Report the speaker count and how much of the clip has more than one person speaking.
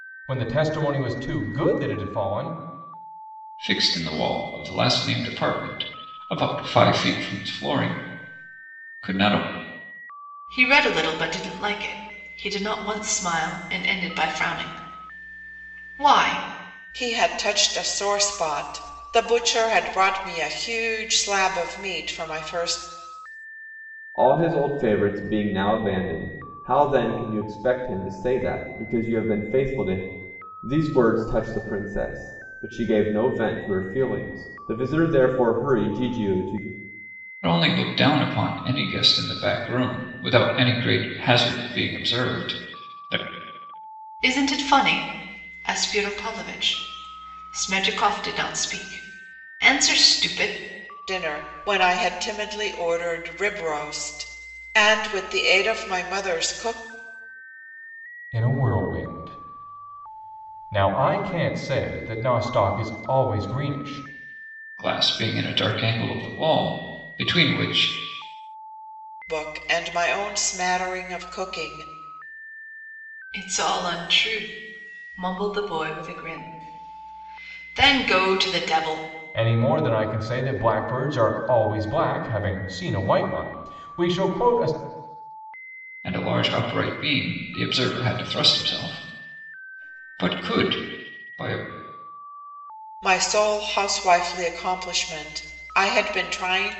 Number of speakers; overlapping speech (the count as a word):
five, no overlap